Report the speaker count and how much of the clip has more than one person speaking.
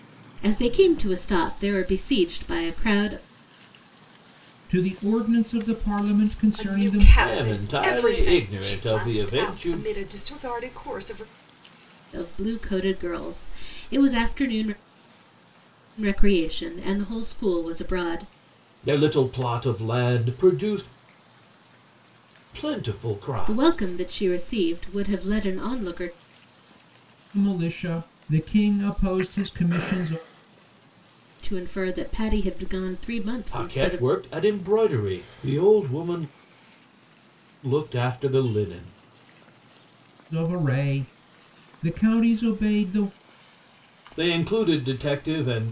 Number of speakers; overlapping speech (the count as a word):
four, about 9%